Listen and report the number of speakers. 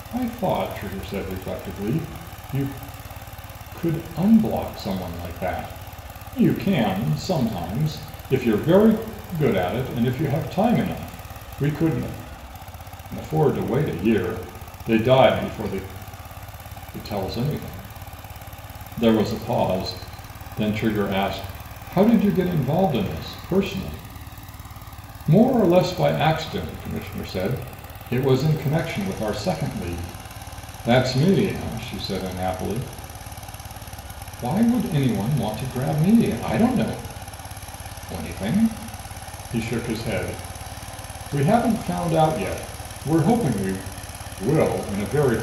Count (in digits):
1